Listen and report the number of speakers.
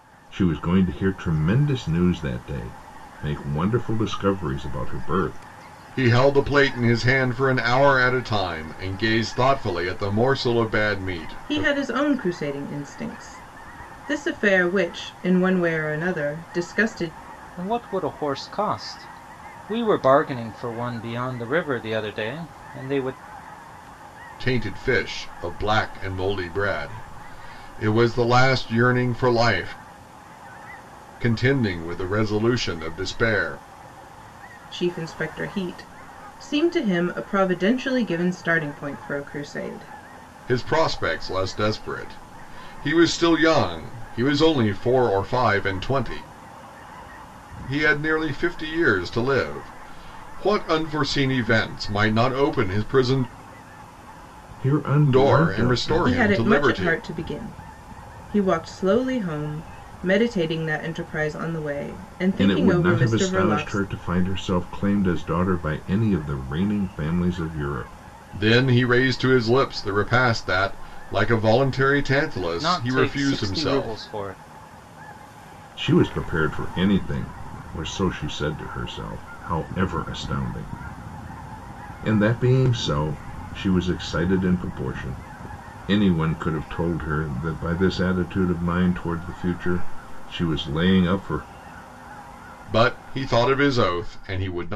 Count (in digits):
4